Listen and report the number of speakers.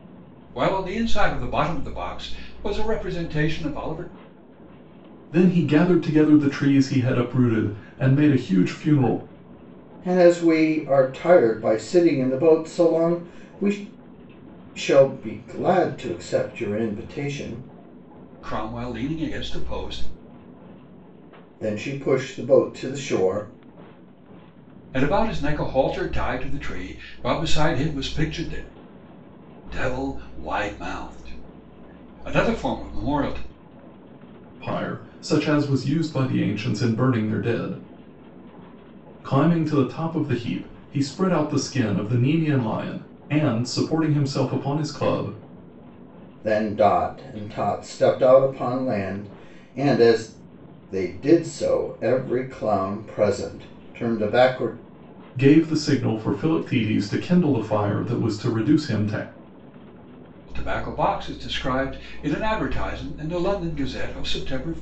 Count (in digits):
3